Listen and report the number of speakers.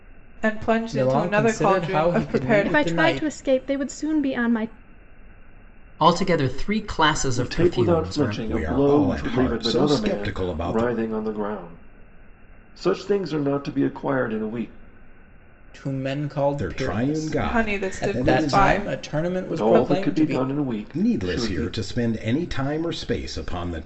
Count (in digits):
6